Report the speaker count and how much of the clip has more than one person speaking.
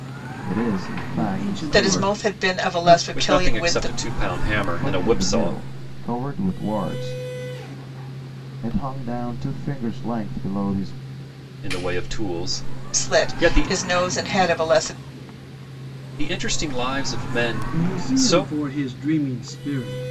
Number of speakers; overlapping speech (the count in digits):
4, about 26%